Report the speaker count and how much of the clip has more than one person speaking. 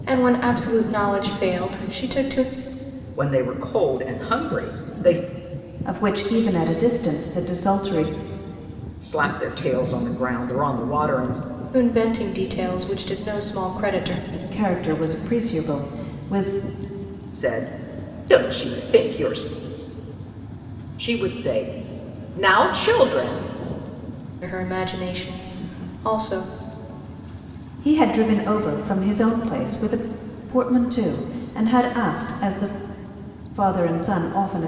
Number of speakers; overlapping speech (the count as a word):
three, no overlap